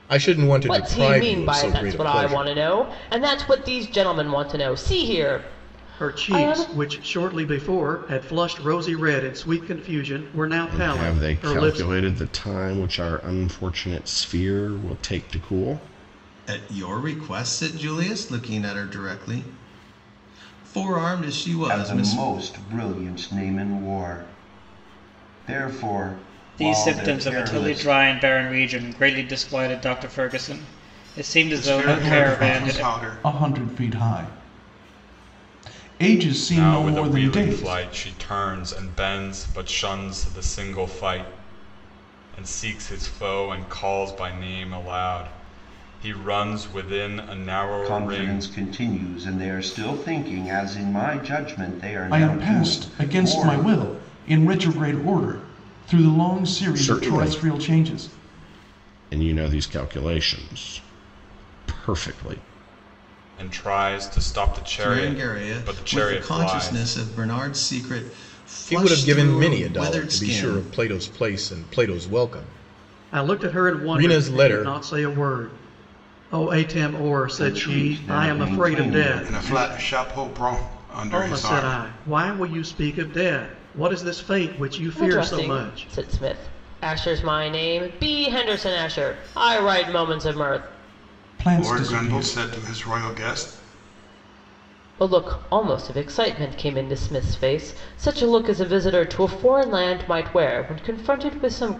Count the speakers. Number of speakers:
ten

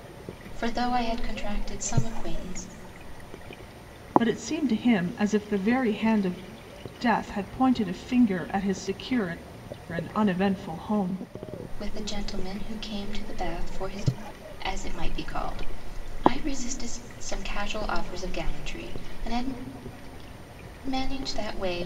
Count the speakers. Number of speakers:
two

